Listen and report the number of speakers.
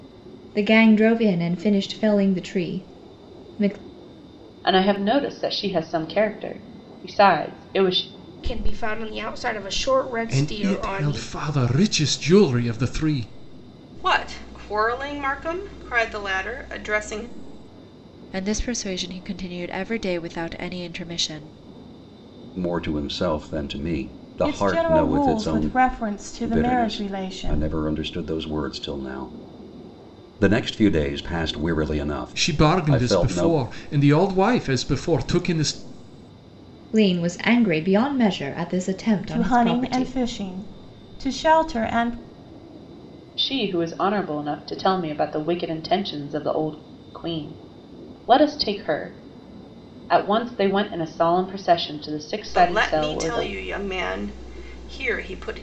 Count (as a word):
eight